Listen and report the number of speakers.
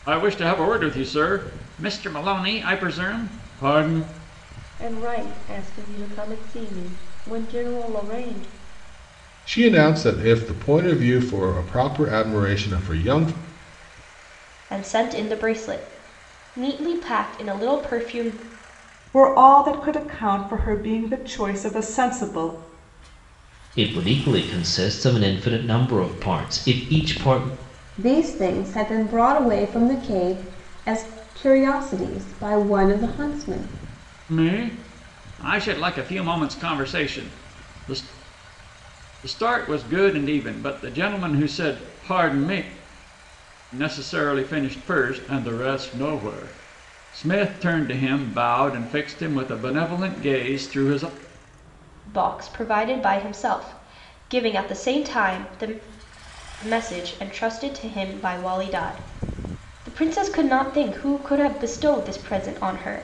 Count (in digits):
7